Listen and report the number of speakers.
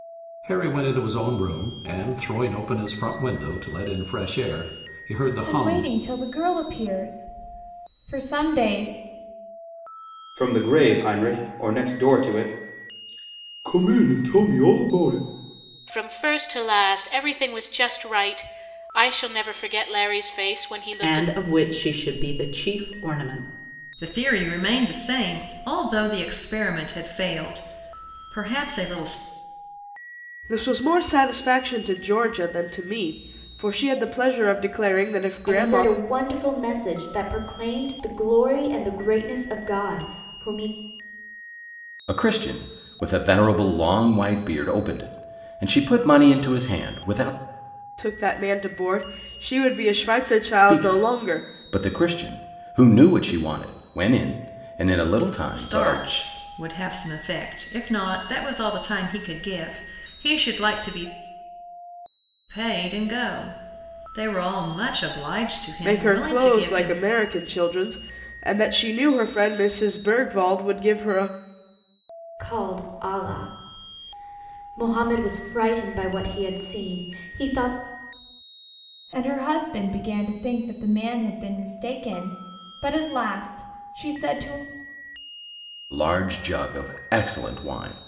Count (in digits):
9